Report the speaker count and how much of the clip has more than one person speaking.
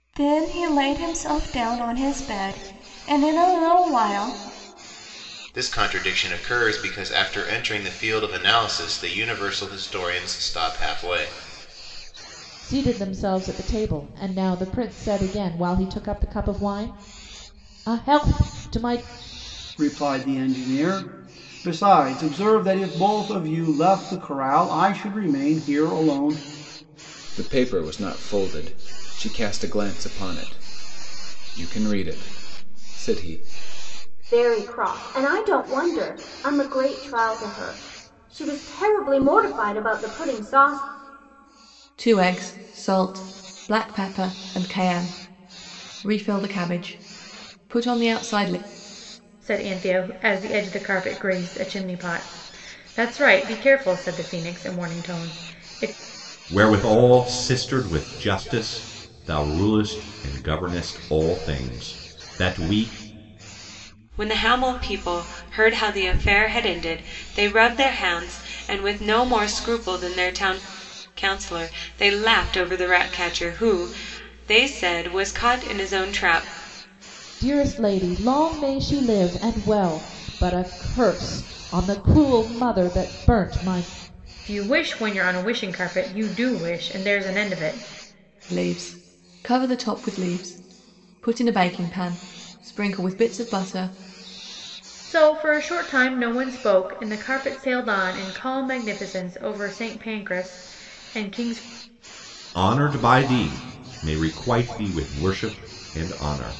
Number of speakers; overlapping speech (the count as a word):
ten, no overlap